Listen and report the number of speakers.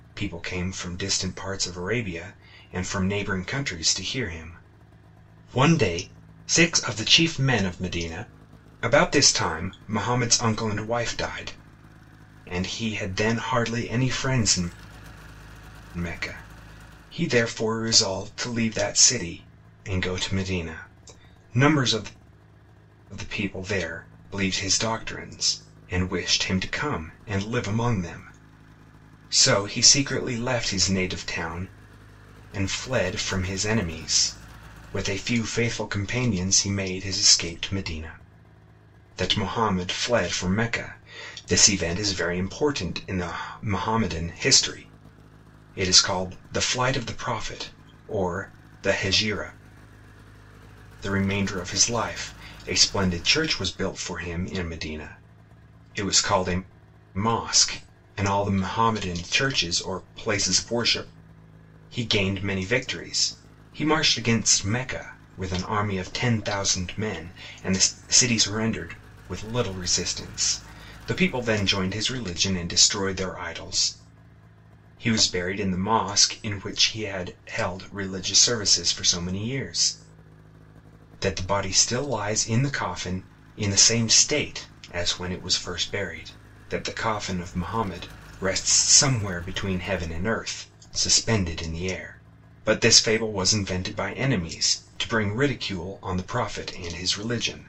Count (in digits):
1